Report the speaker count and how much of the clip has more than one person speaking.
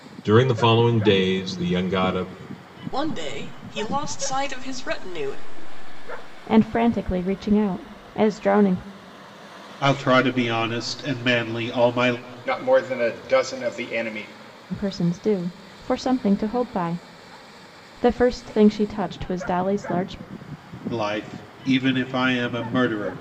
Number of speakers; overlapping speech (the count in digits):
5, no overlap